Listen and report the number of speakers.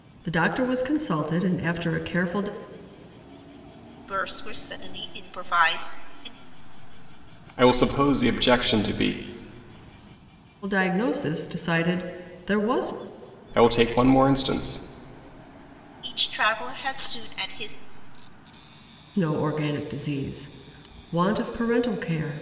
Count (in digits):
3